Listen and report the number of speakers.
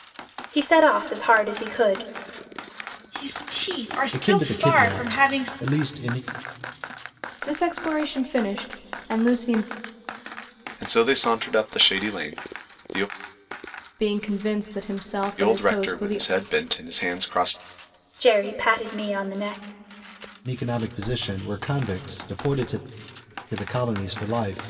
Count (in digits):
5